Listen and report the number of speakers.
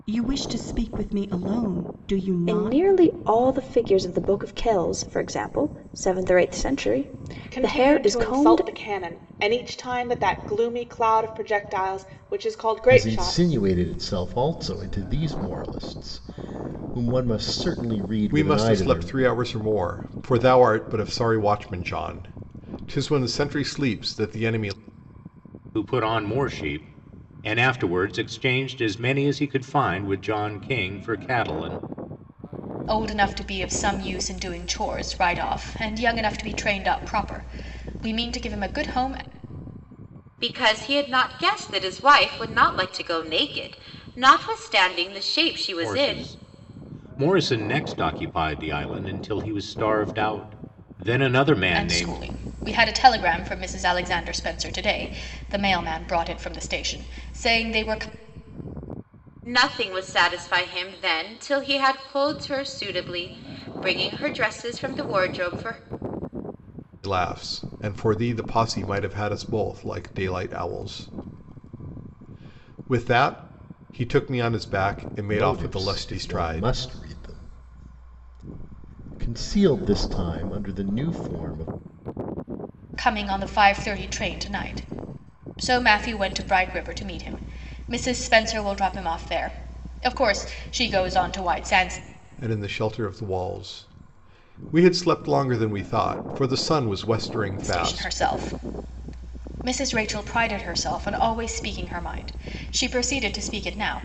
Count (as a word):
eight